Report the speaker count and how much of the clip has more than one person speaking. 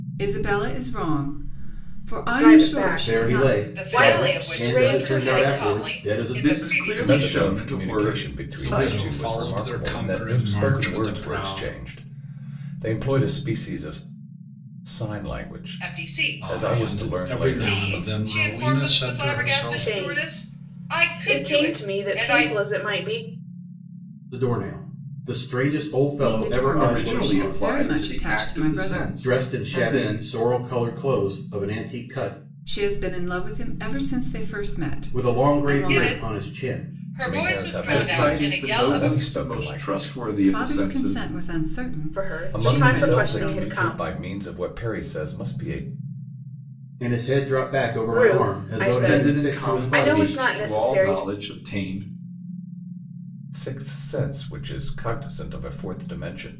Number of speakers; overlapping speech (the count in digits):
7, about 55%